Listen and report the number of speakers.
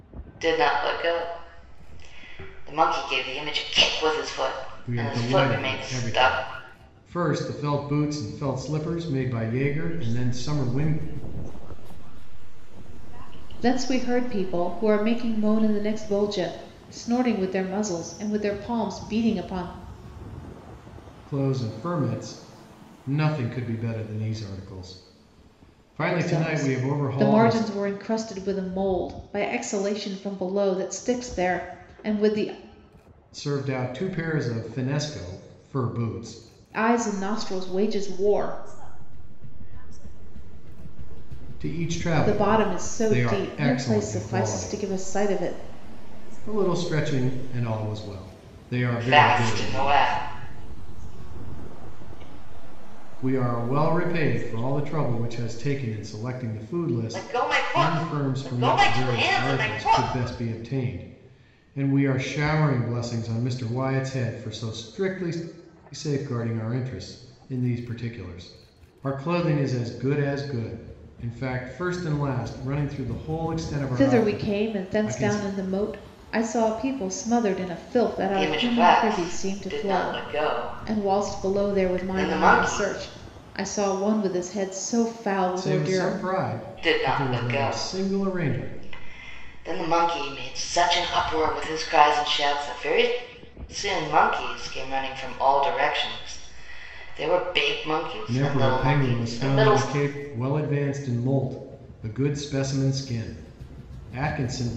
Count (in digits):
4